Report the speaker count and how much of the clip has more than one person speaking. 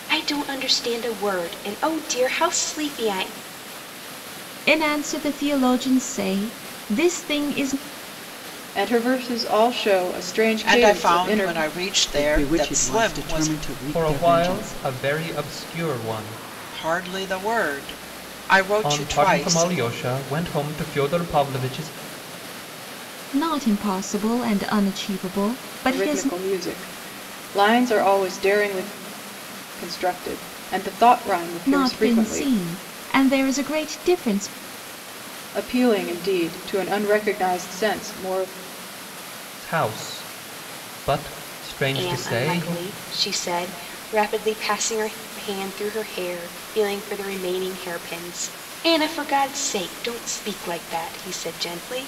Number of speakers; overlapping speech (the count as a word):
six, about 12%